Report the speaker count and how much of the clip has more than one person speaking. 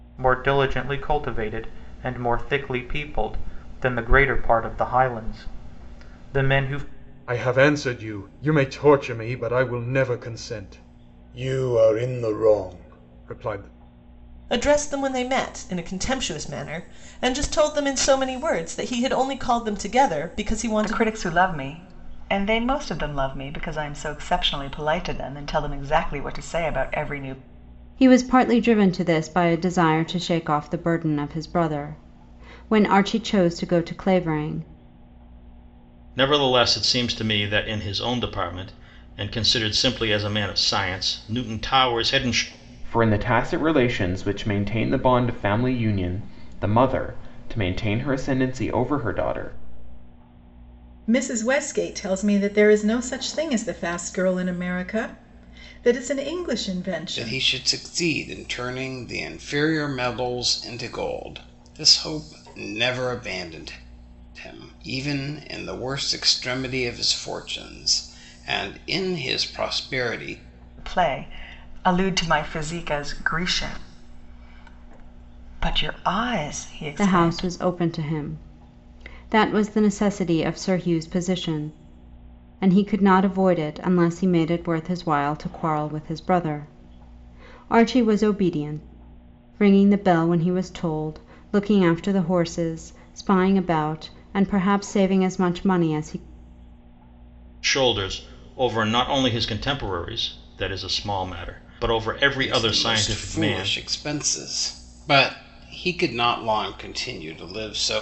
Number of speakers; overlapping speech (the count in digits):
9, about 2%